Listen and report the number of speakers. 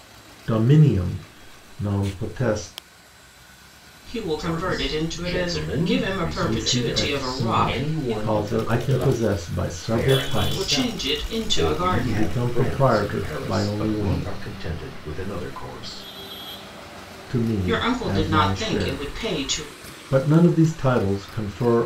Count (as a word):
three